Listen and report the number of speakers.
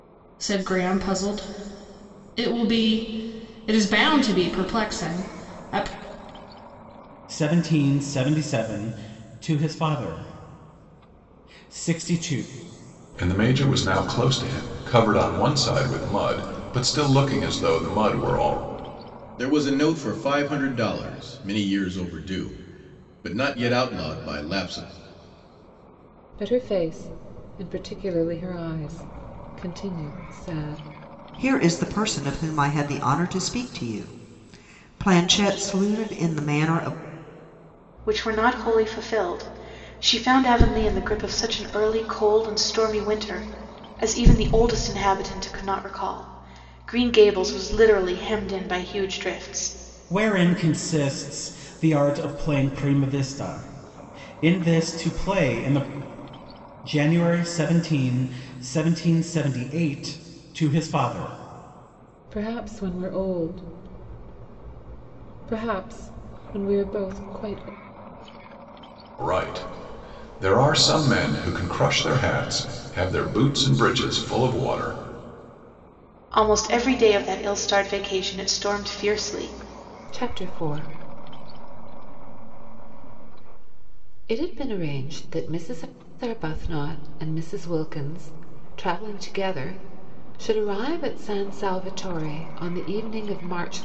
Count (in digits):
7